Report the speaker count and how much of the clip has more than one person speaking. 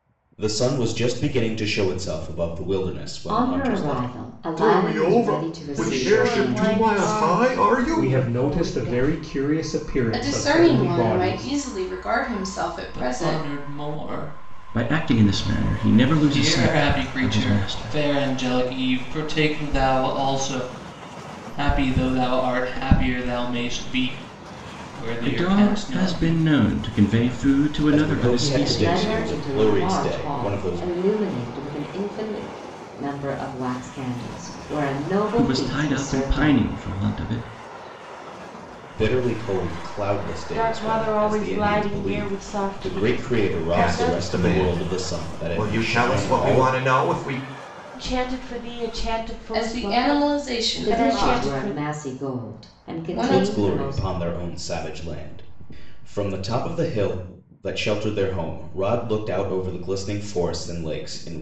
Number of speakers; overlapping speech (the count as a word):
eight, about 45%